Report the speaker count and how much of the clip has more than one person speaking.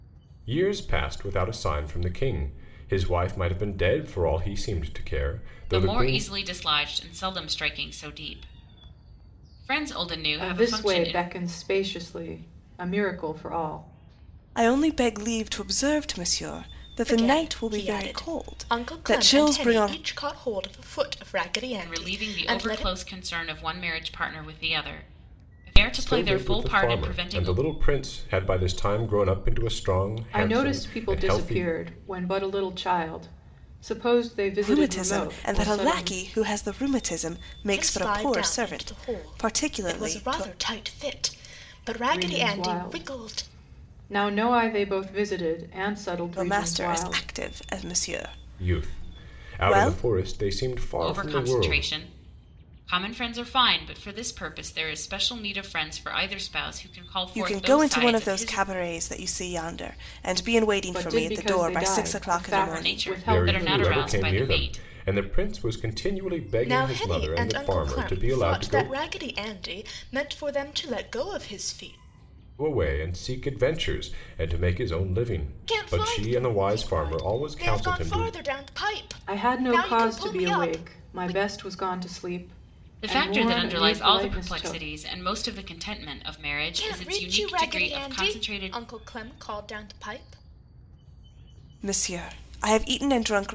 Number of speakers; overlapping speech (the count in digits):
5, about 36%